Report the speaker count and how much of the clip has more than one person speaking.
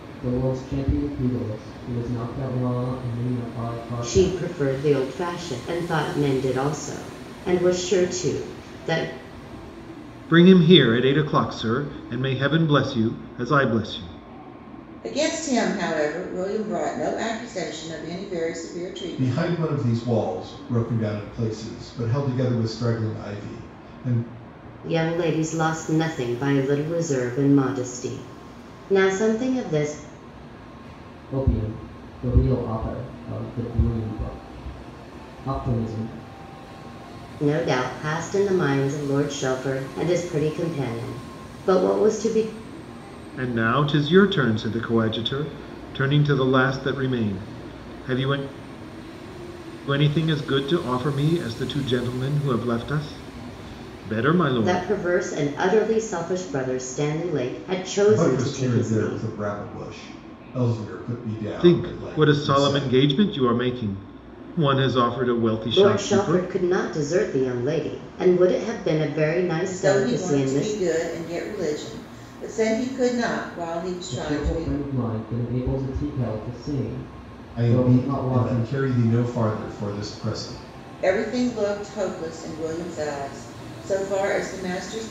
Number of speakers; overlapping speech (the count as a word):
five, about 9%